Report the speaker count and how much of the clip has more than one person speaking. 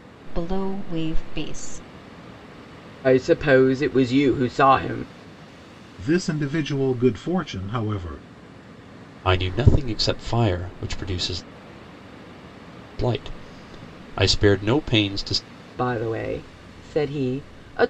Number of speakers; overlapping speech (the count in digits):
4, no overlap